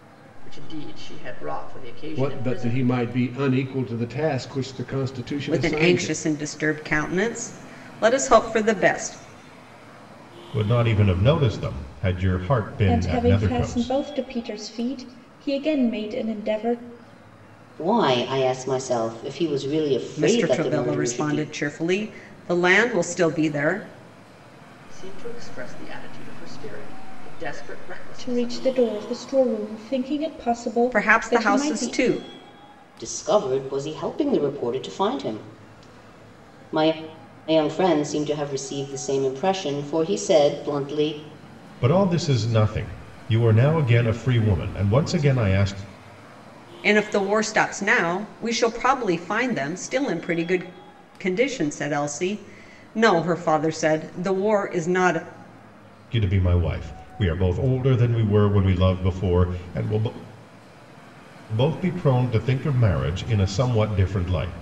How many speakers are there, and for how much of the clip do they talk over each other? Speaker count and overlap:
6, about 9%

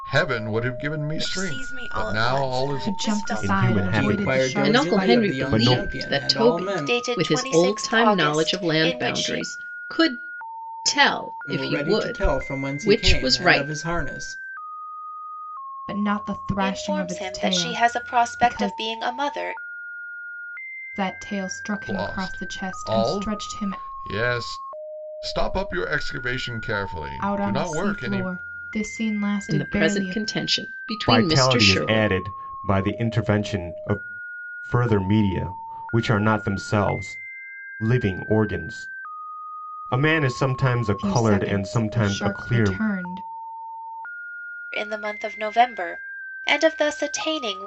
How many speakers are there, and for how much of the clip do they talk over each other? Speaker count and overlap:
7, about 41%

